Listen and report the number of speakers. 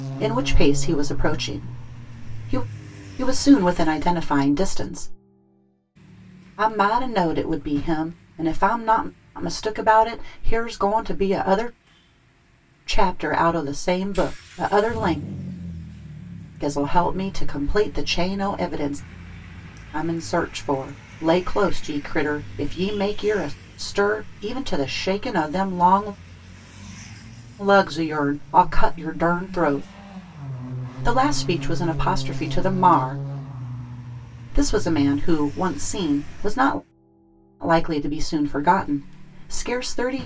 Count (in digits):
1